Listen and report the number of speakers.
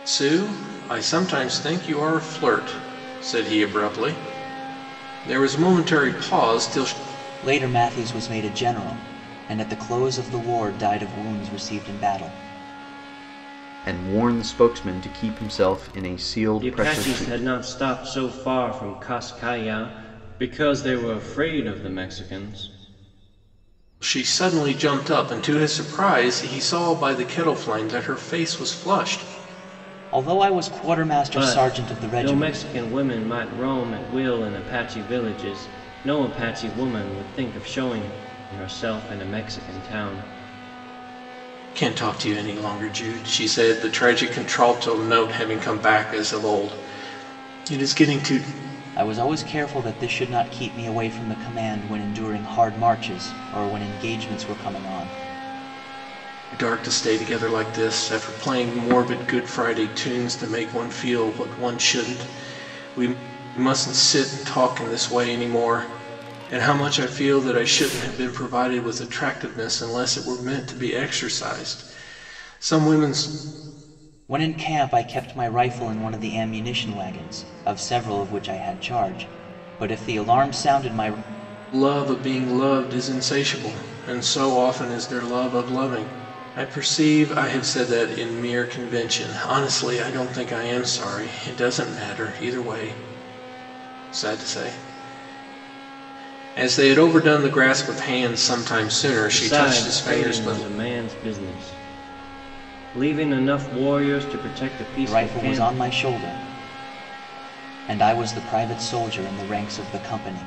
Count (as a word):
four